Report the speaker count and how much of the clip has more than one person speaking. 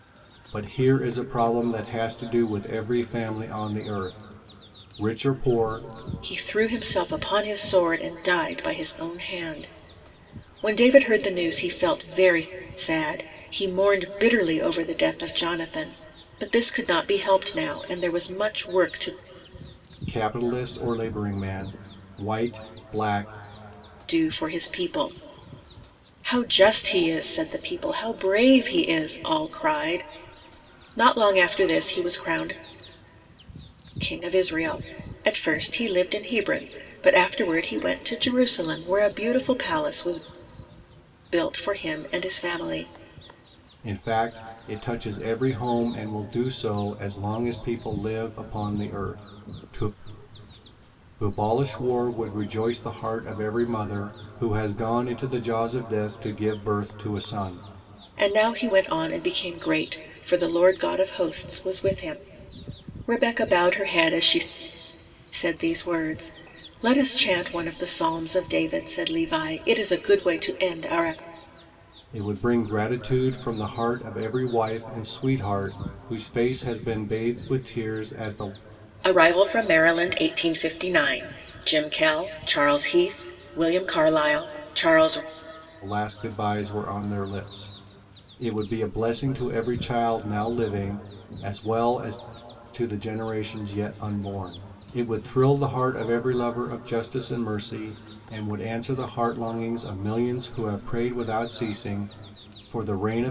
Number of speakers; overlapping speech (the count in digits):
2, no overlap